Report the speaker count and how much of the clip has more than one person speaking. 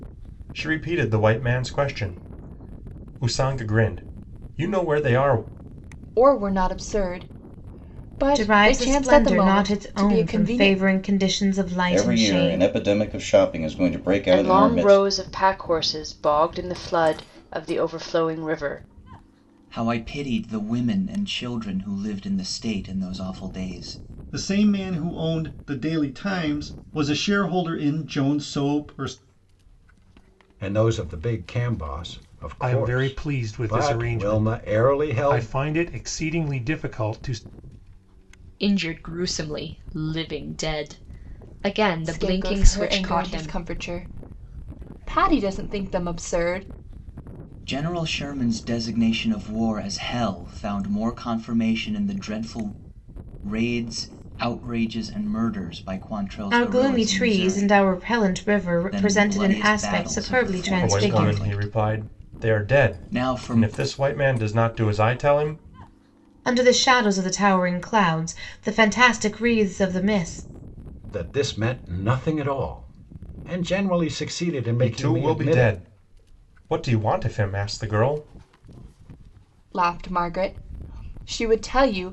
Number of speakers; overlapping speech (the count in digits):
10, about 19%